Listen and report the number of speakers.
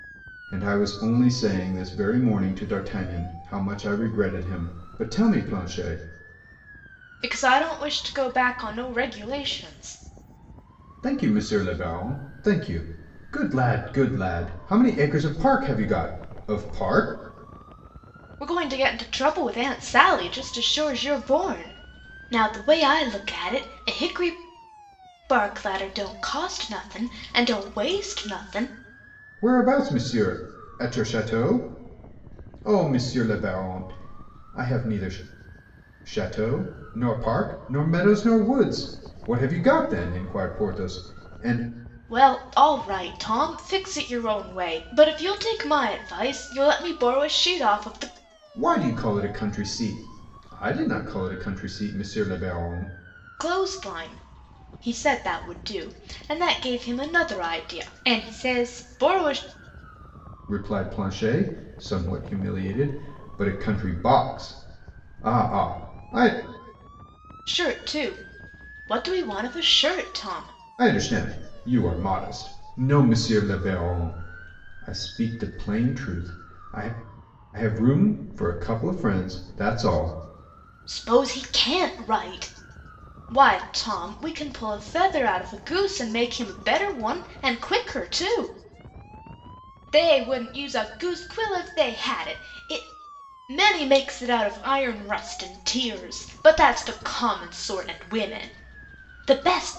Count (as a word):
two